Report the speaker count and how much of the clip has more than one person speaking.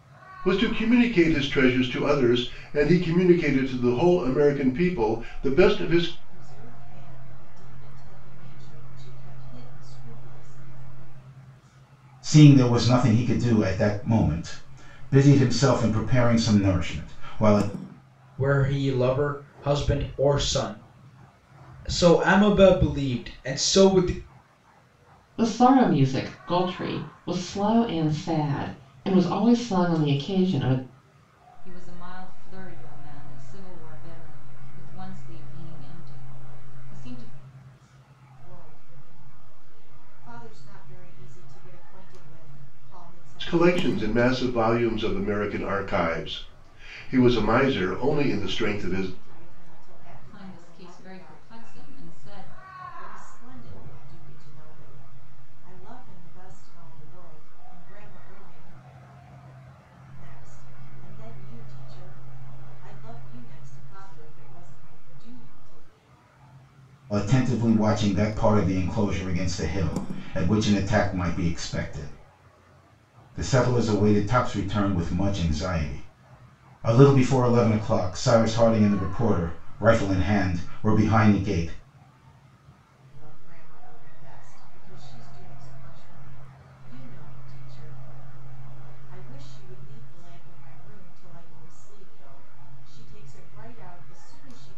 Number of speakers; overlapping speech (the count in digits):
6, about 4%